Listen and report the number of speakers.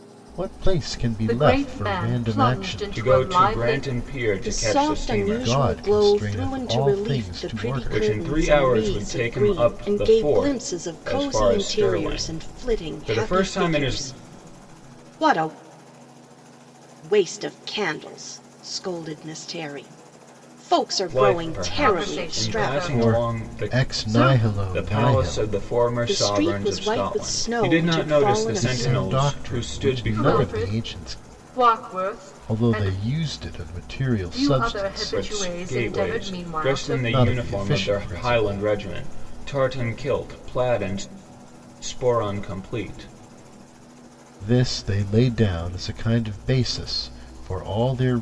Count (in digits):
4